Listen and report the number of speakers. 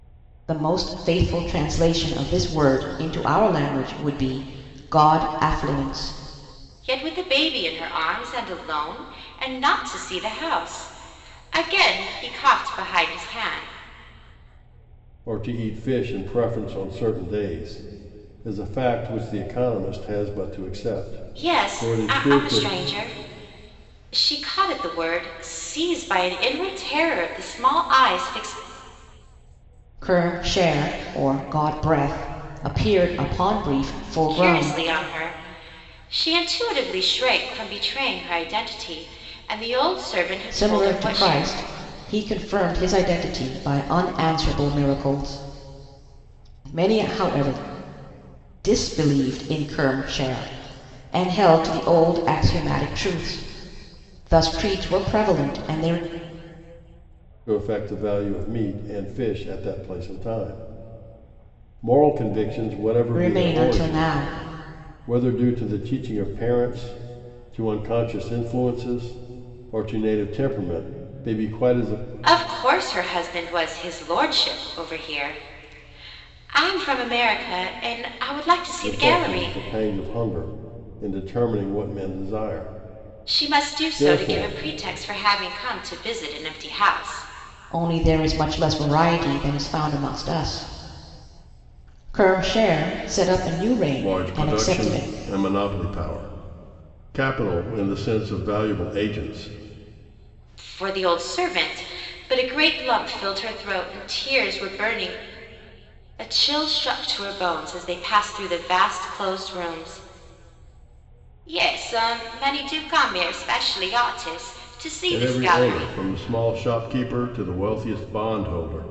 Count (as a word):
three